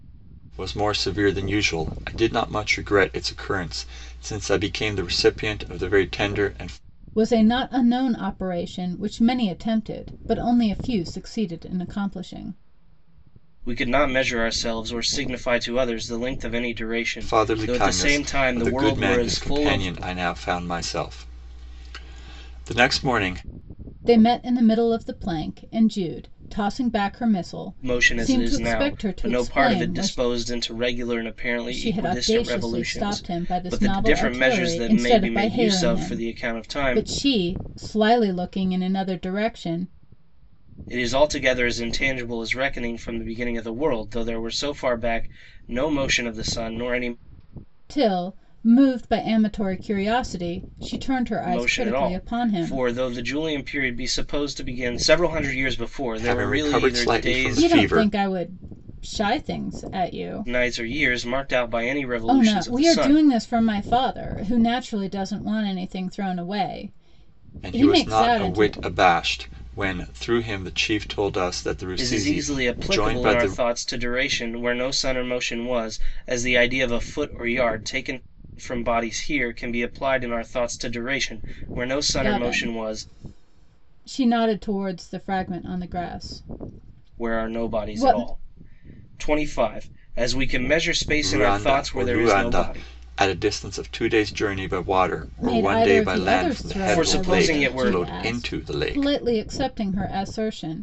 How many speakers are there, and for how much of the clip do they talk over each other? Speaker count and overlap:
three, about 27%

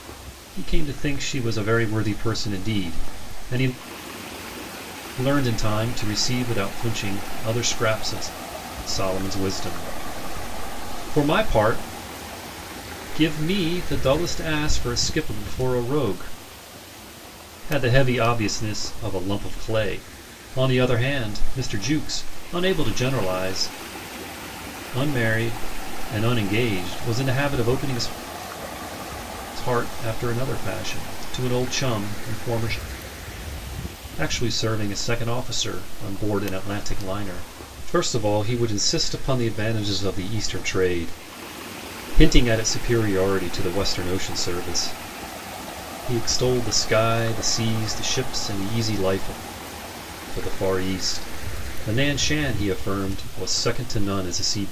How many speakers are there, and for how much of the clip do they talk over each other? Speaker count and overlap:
one, no overlap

